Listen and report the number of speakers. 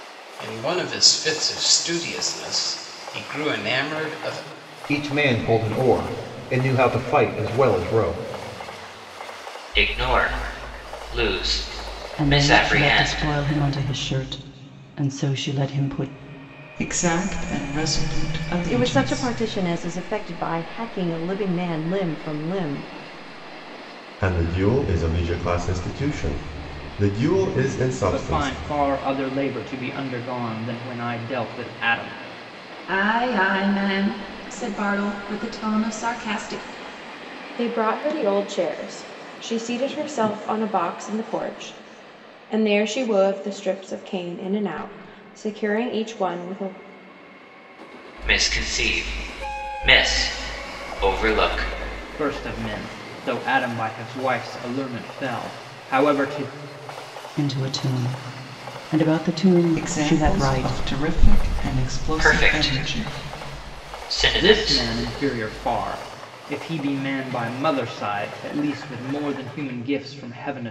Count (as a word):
ten